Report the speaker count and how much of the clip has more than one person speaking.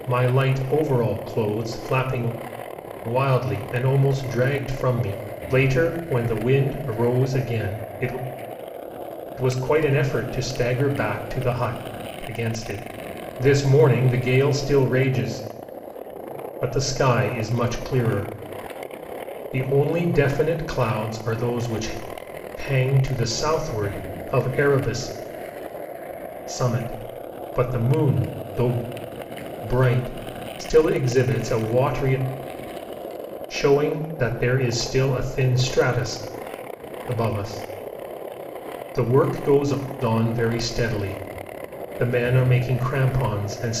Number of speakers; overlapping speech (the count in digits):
1, no overlap